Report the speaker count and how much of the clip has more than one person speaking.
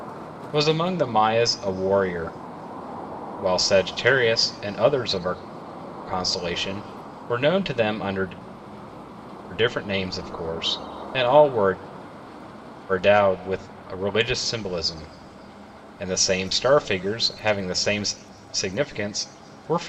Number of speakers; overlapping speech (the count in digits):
1, no overlap